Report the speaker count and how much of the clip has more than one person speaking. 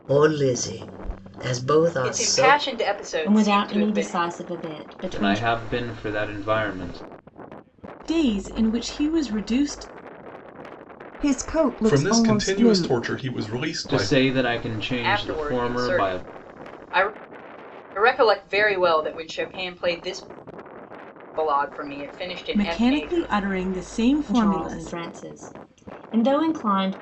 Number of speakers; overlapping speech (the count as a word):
seven, about 23%